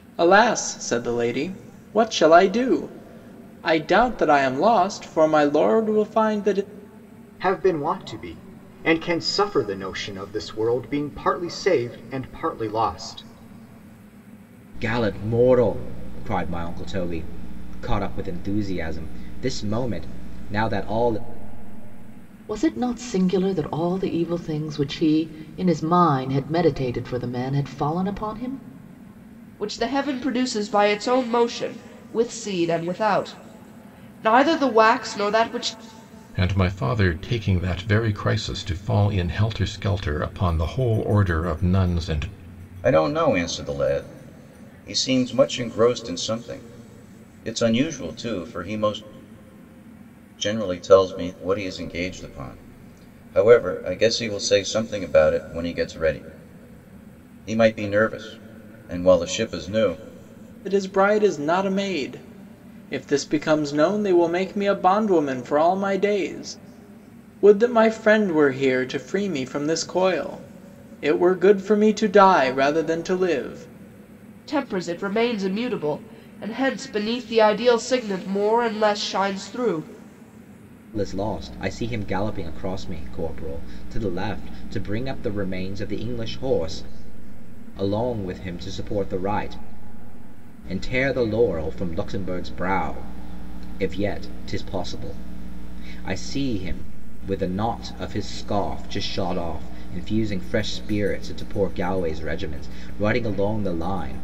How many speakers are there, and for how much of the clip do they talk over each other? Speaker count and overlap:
seven, no overlap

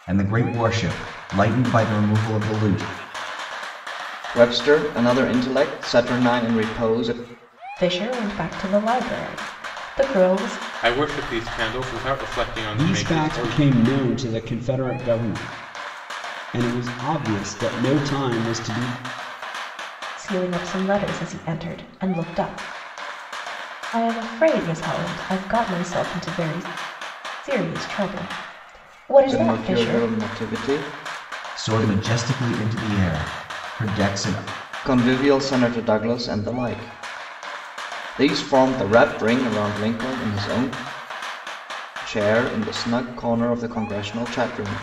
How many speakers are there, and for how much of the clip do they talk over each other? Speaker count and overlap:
five, about 5%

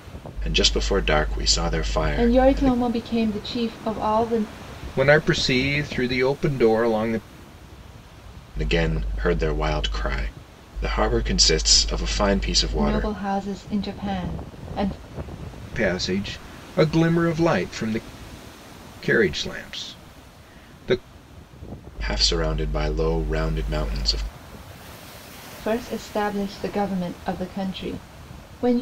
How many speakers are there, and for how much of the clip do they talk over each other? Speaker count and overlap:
three, about 3%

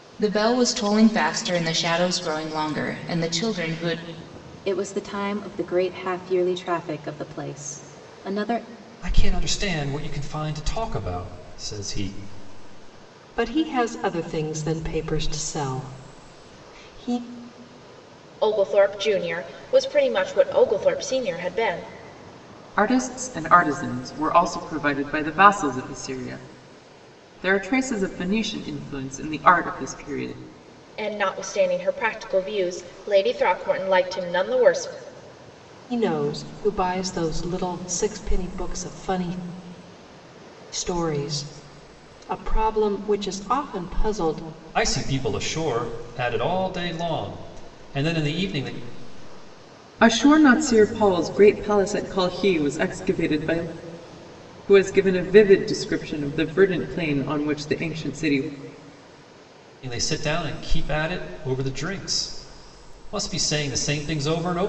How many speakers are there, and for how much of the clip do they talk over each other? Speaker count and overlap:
six, no overlap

